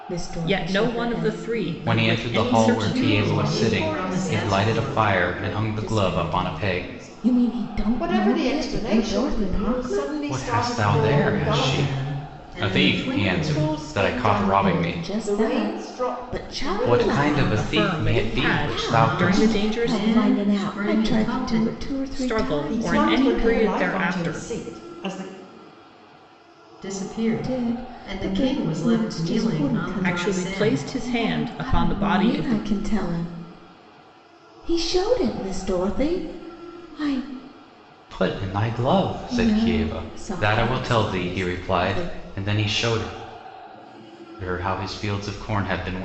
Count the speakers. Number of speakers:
5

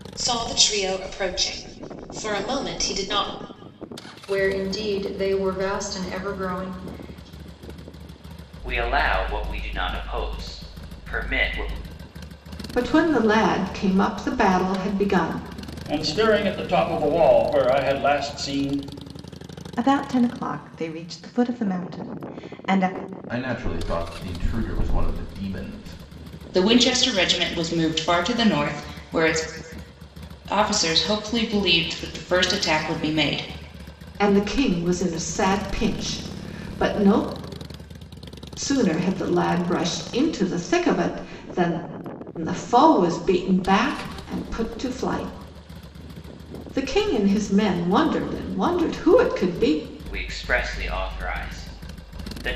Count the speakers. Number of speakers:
8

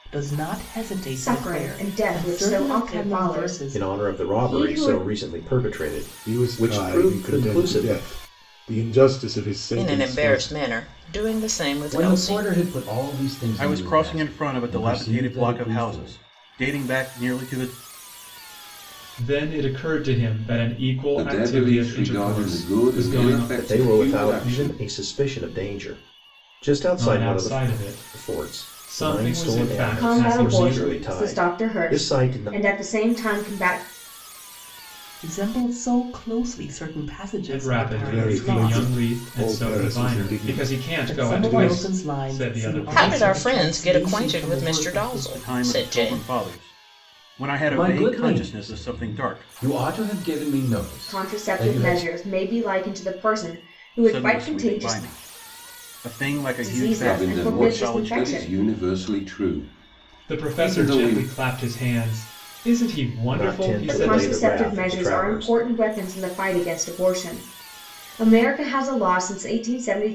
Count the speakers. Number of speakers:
9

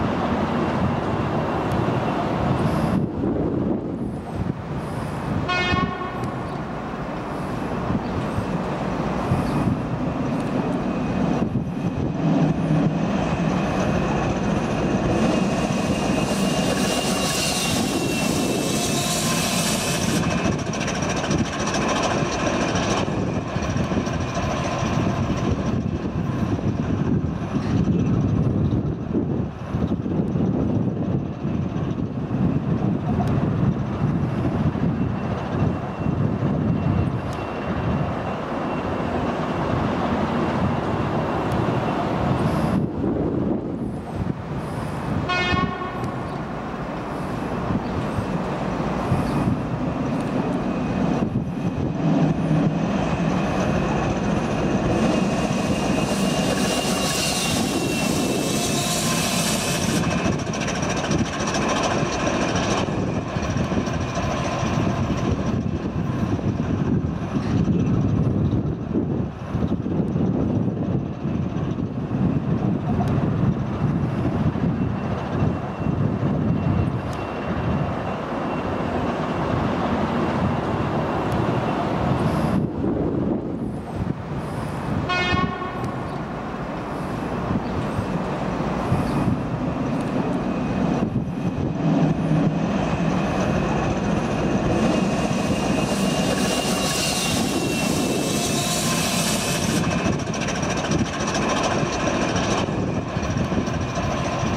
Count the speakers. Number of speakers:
0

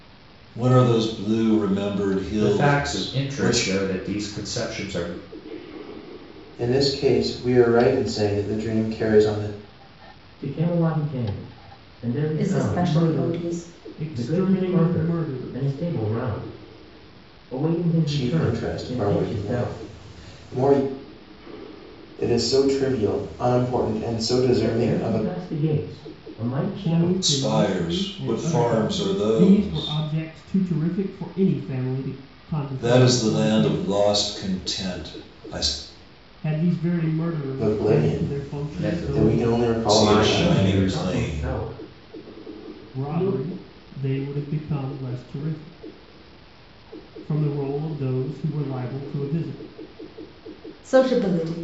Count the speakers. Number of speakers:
6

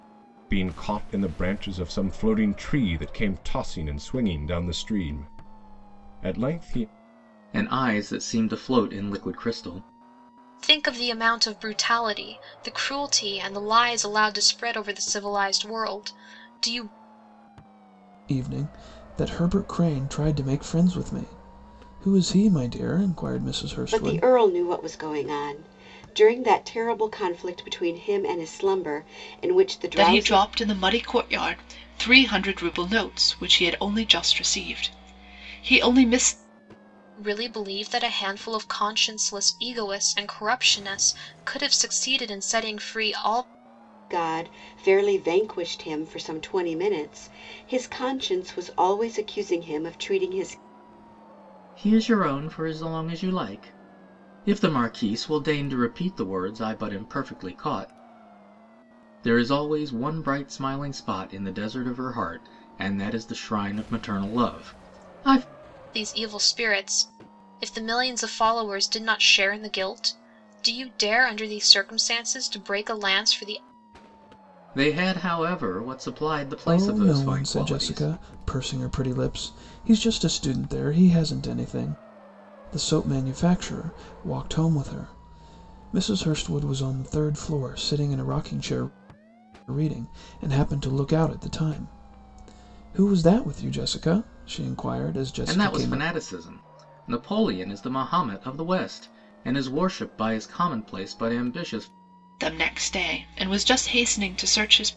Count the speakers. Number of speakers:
6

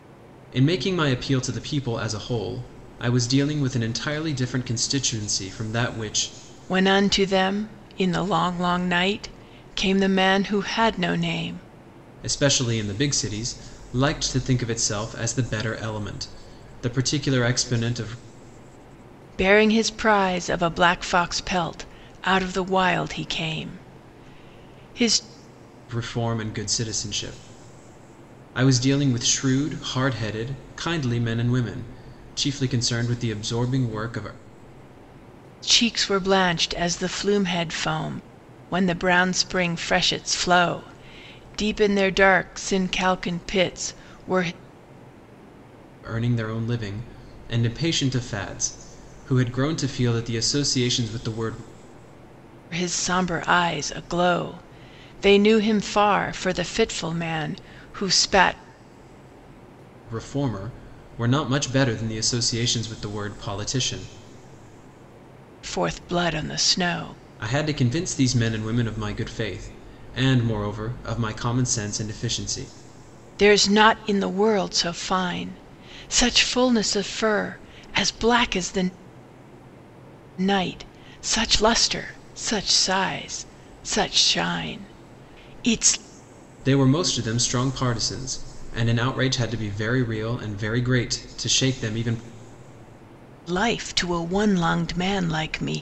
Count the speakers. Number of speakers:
2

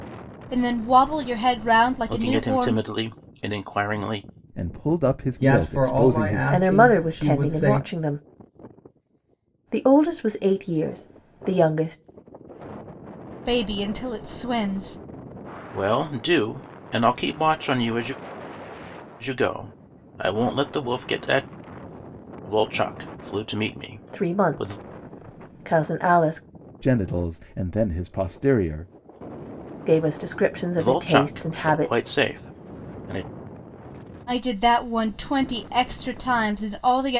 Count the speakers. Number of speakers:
5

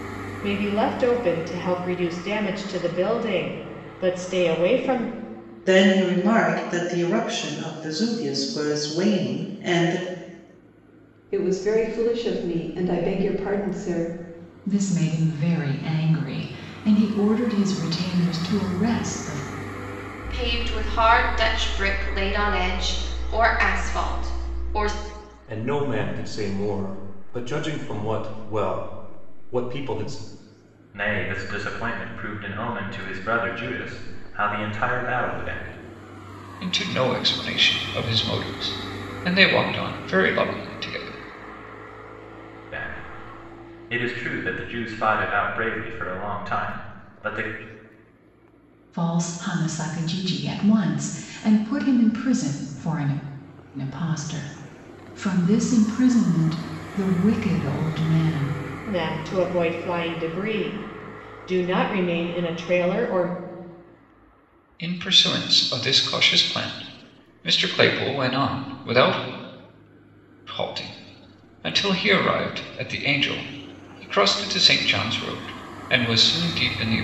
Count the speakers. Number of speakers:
8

